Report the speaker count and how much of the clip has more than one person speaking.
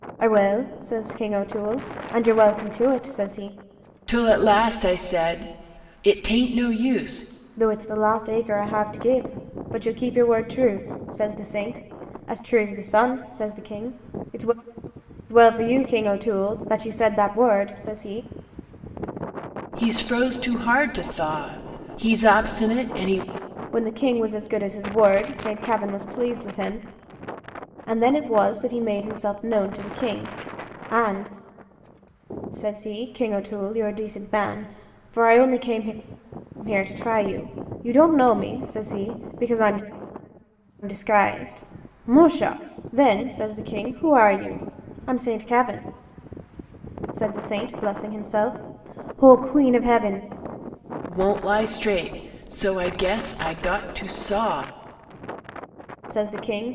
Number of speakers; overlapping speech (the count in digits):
2, no overlap